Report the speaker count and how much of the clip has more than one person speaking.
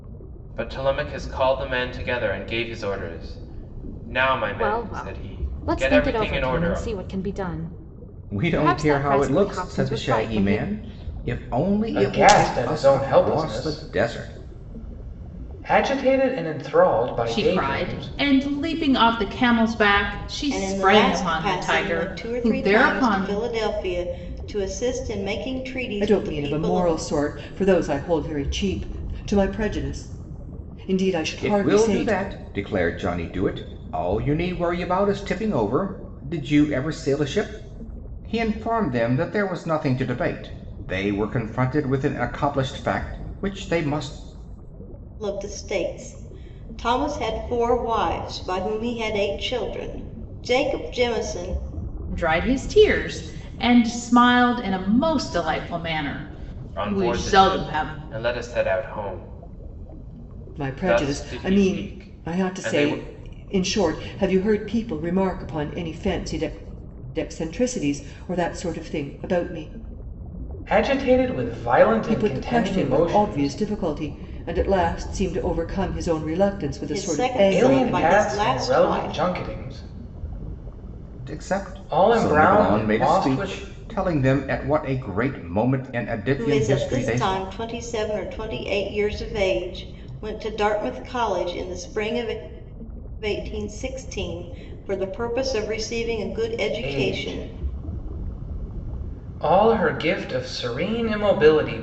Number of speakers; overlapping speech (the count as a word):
seven, about 24%